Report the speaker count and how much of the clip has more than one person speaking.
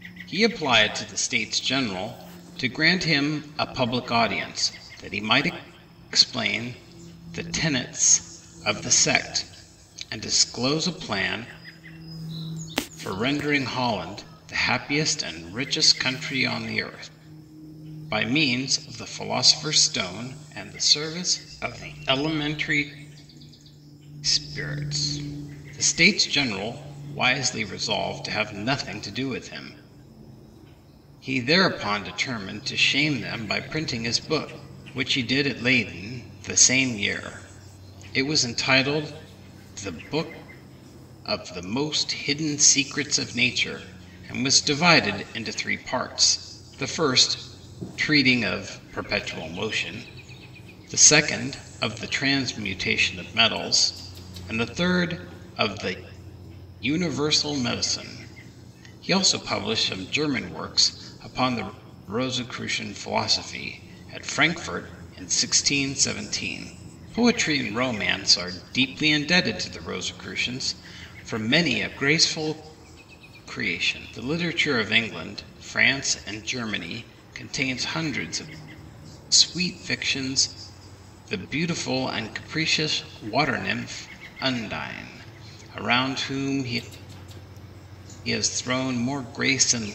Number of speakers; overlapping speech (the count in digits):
1, no overlap